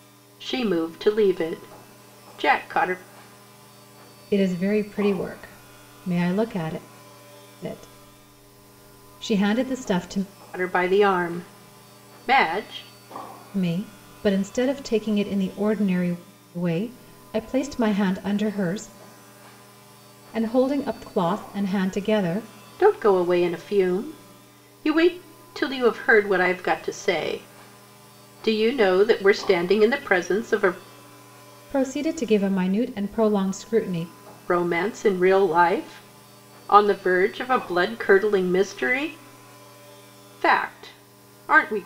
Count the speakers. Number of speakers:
2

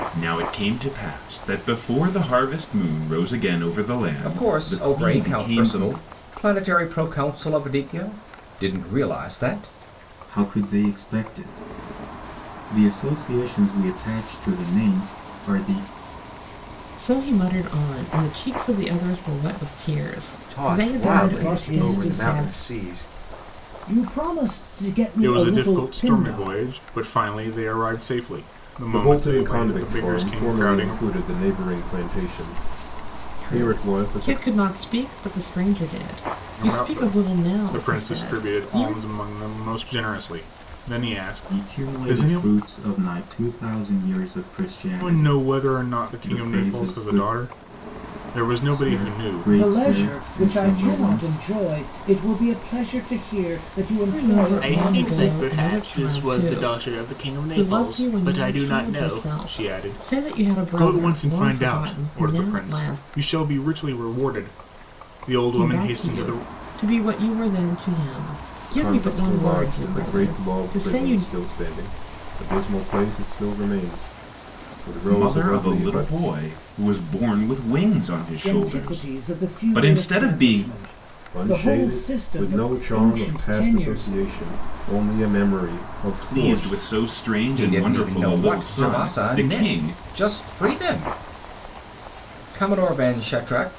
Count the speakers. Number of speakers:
8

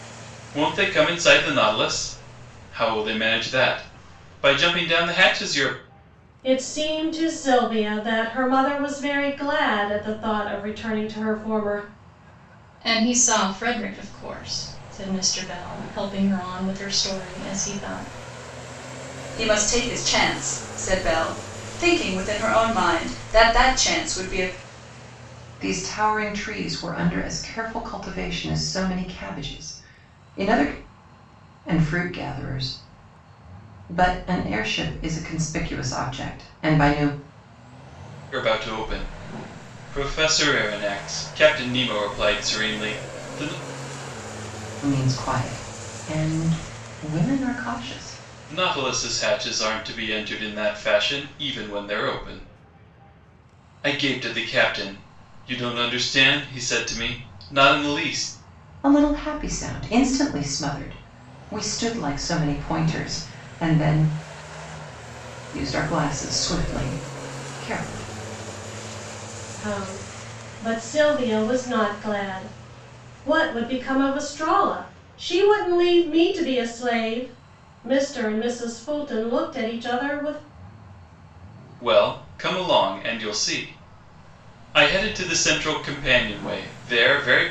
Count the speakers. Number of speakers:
5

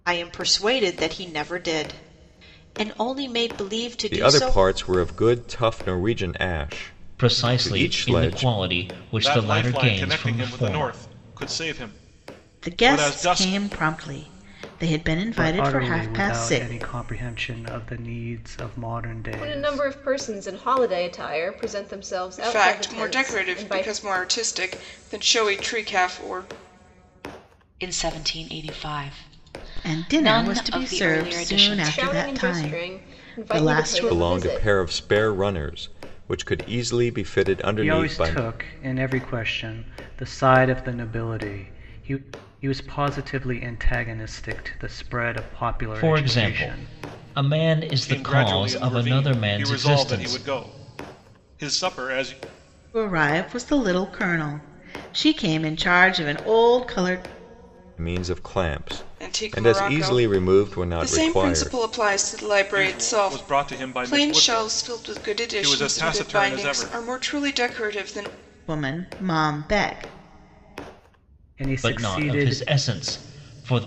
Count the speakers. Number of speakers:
9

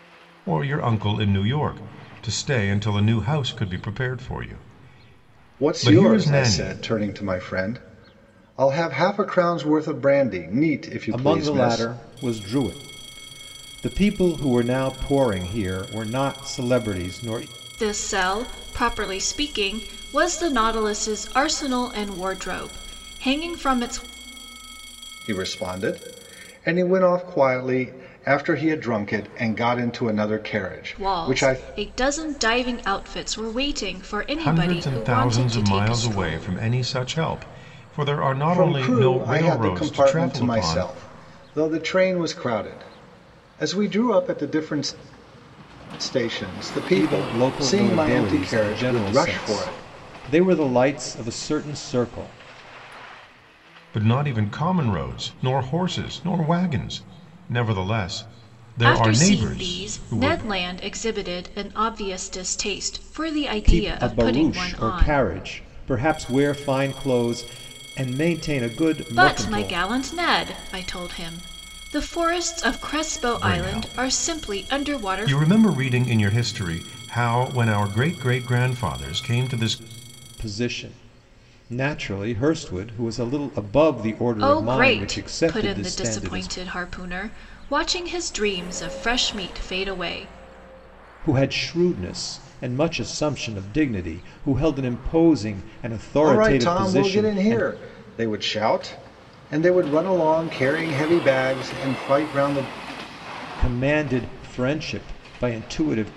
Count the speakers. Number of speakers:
4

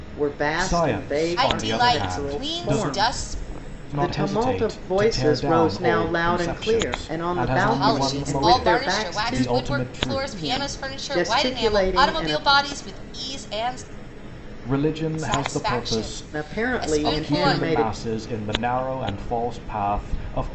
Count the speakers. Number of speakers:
3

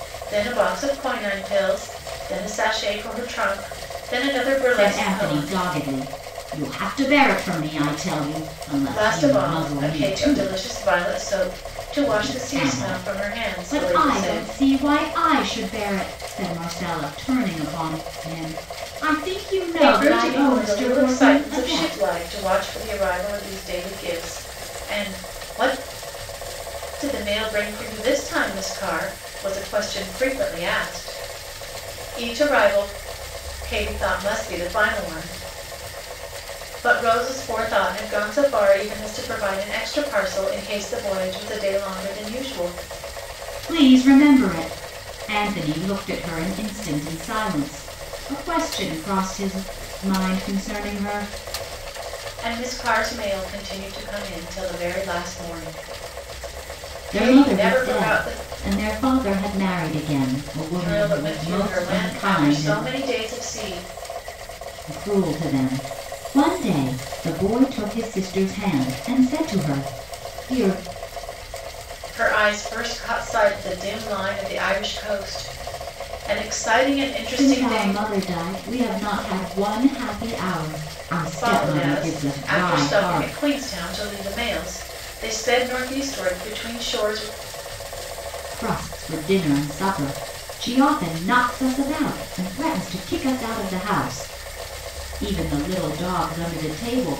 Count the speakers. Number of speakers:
2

